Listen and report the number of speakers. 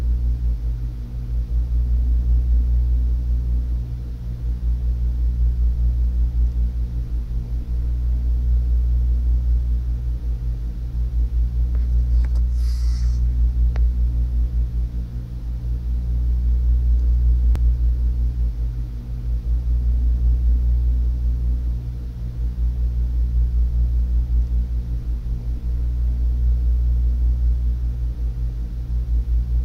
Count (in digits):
0